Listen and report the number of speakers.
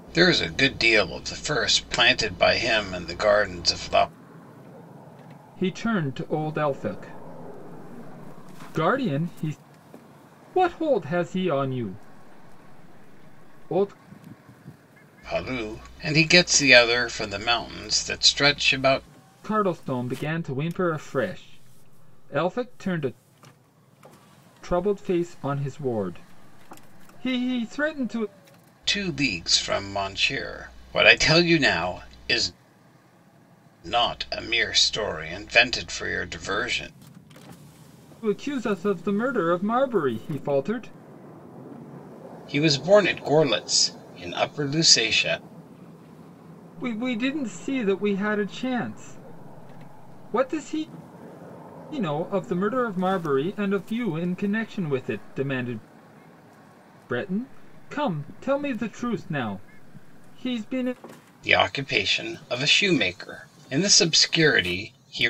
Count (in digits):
2